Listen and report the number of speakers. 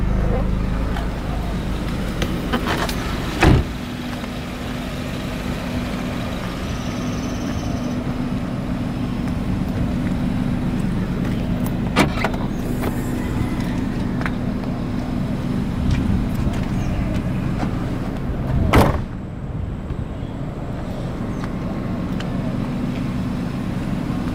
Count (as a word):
zero